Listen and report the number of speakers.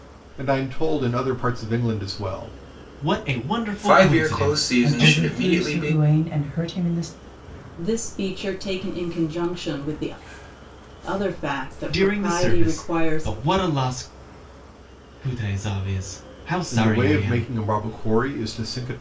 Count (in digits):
5